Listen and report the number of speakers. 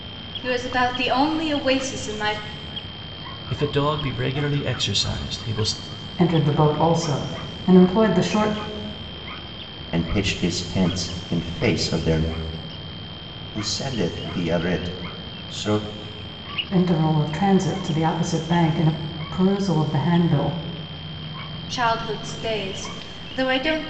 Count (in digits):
4